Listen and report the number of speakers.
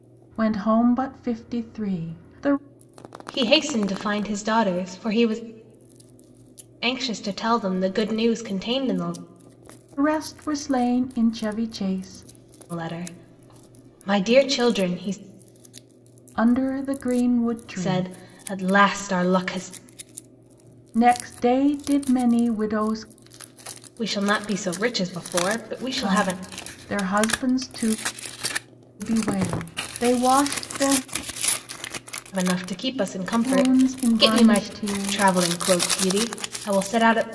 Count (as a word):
two